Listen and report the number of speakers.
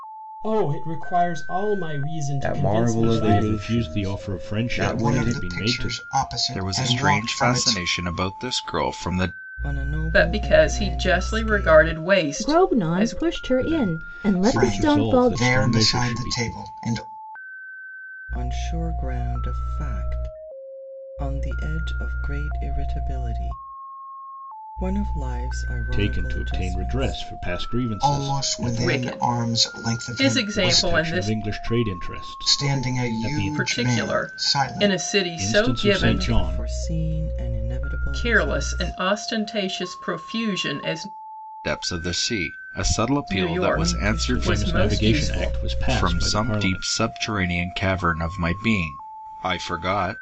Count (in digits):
8